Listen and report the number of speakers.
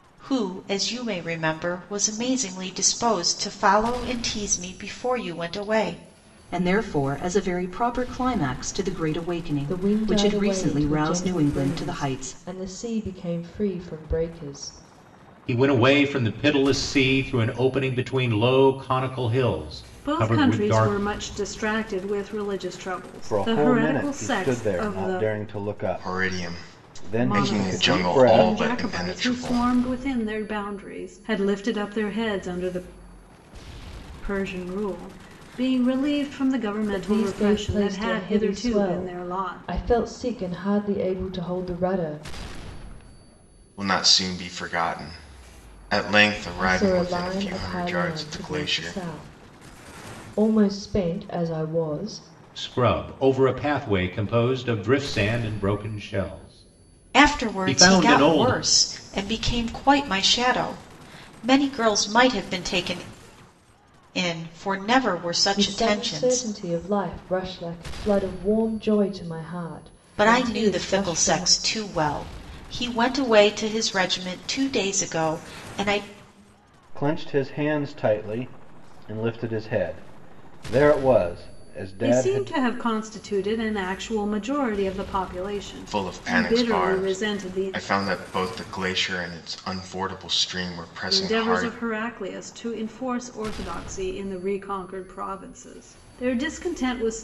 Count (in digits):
7